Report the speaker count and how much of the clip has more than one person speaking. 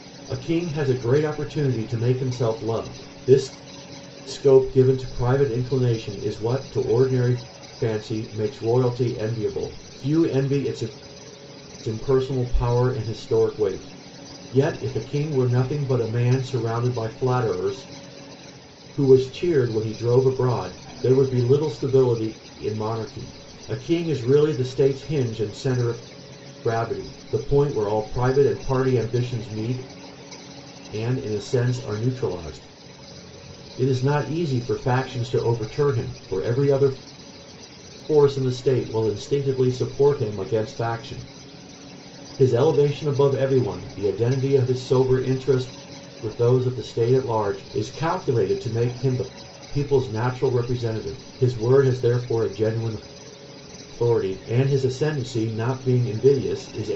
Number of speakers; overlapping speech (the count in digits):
1, no overlap